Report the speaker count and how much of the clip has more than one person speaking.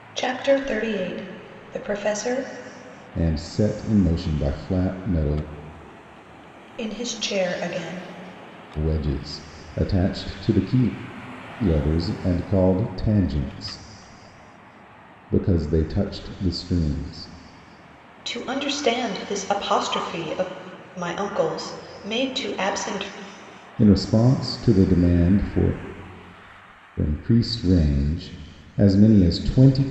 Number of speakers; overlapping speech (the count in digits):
2, no overlap